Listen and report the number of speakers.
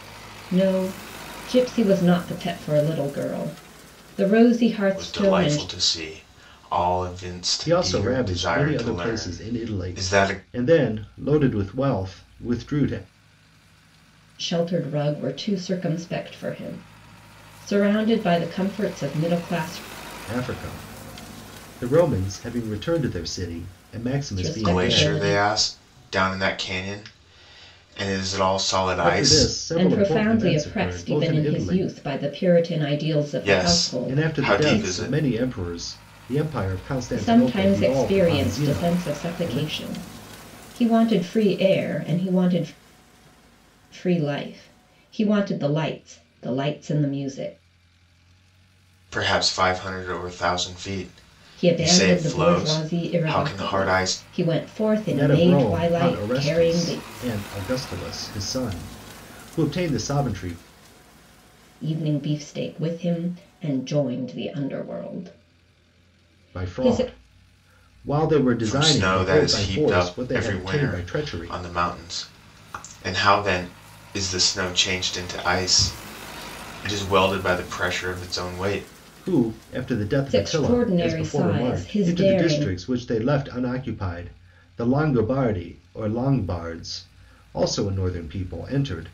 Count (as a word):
three